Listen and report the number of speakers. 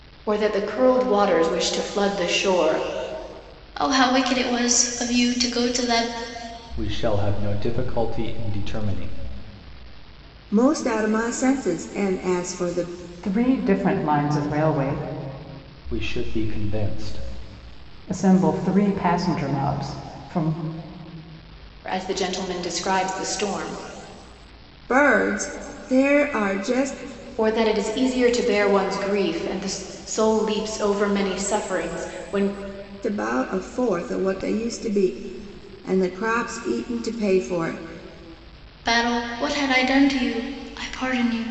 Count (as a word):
five